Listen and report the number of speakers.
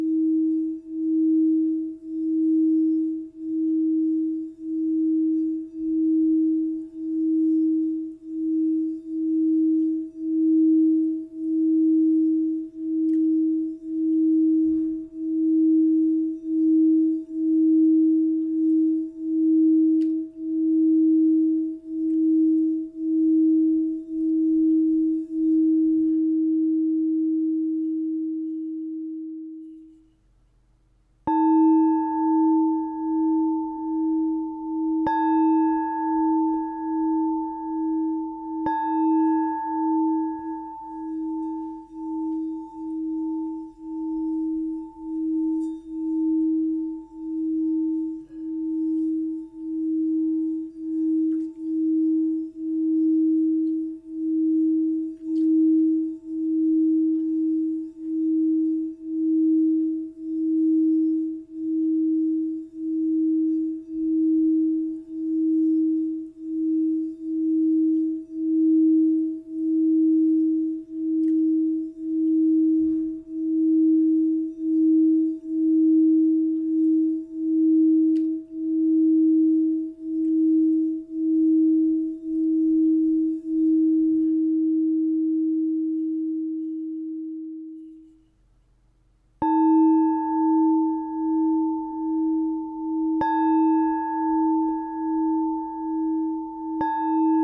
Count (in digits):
0